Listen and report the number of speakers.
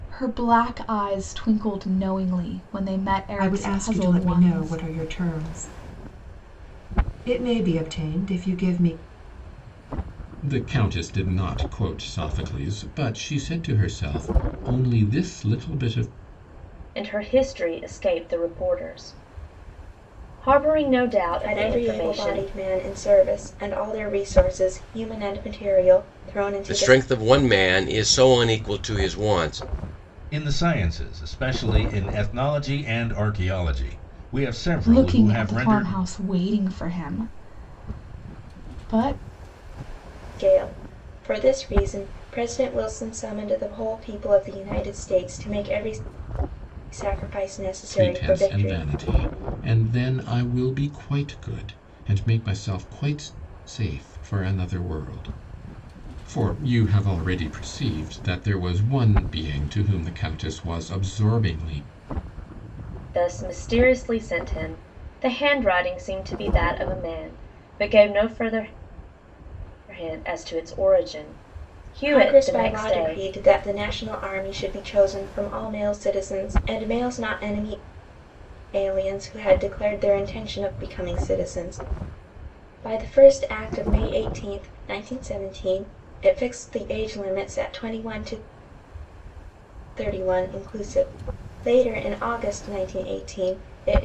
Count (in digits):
7